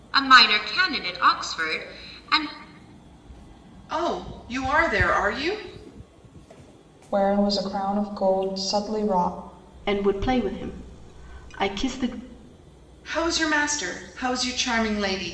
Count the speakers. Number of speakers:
4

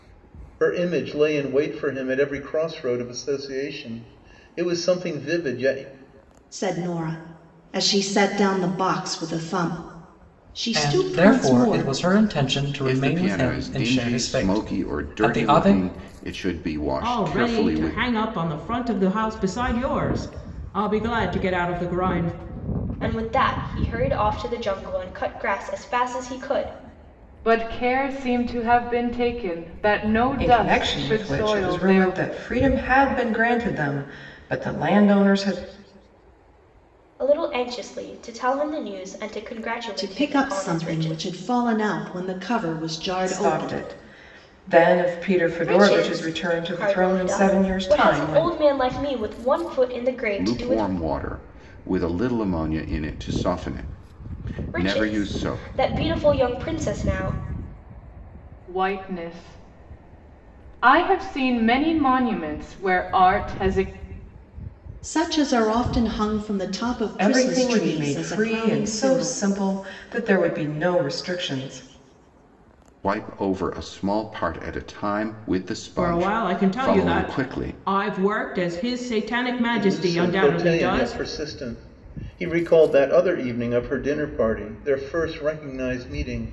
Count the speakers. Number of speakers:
8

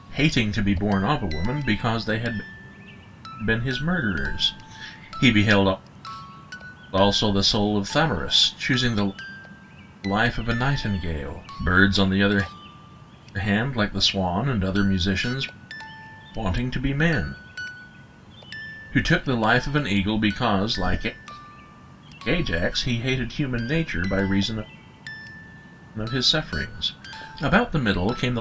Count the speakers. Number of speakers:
1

